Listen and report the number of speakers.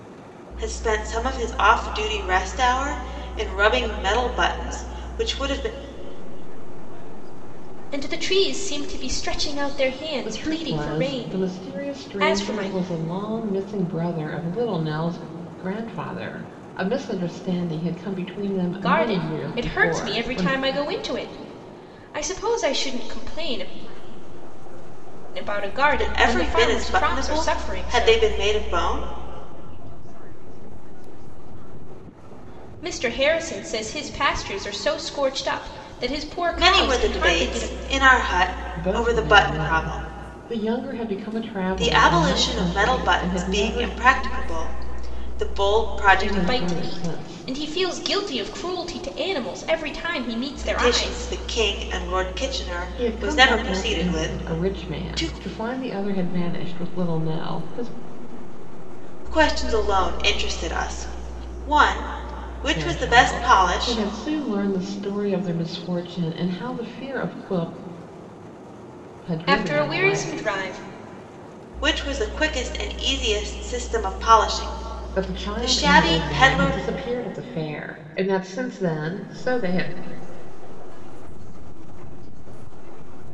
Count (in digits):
4